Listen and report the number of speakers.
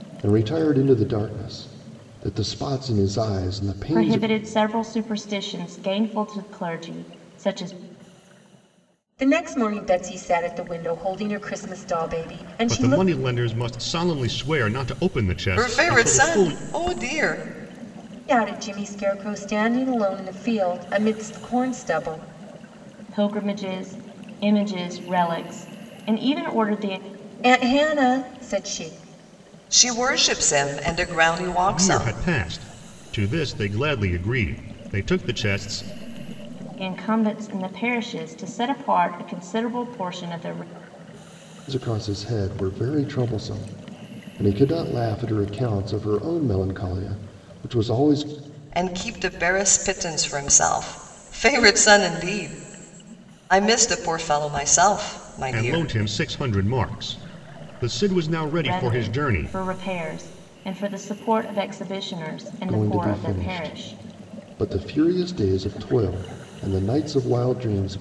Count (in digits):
5